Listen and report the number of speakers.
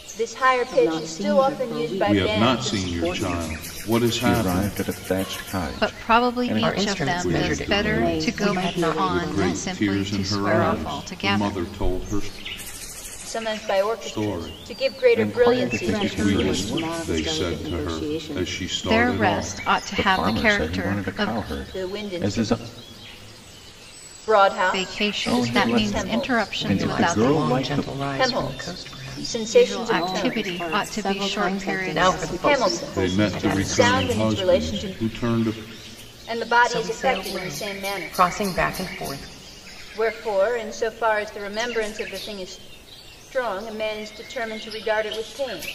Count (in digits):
6